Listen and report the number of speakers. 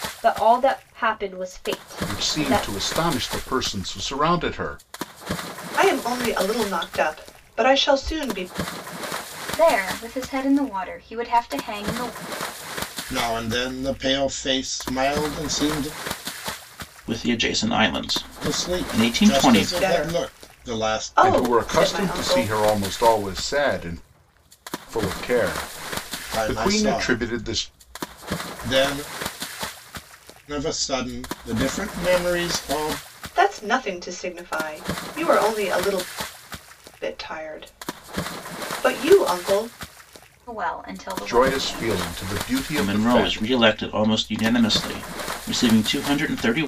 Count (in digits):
6